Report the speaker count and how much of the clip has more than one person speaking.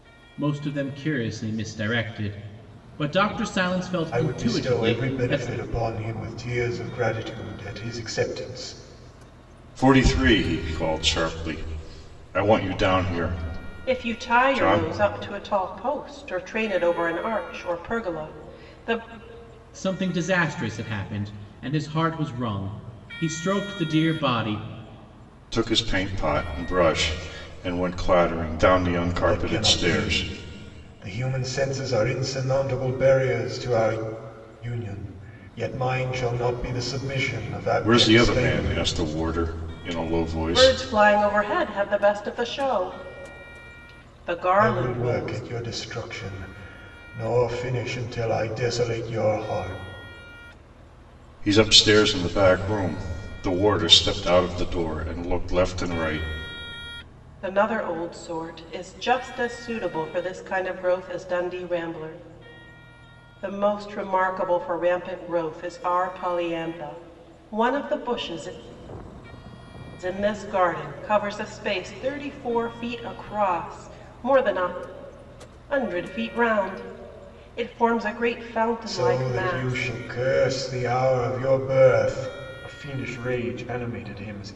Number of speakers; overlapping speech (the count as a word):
four, about 8%